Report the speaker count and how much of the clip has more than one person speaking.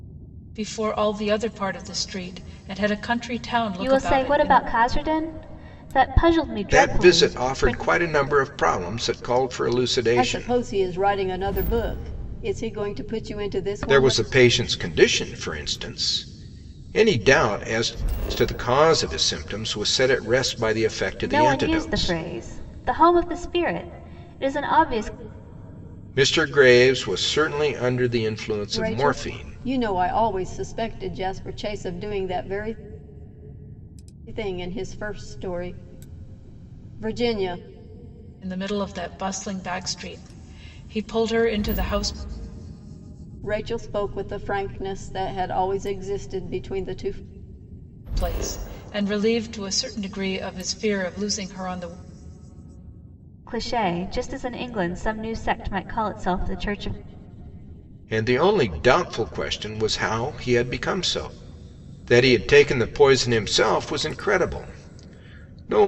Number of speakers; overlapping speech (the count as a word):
four, about 7%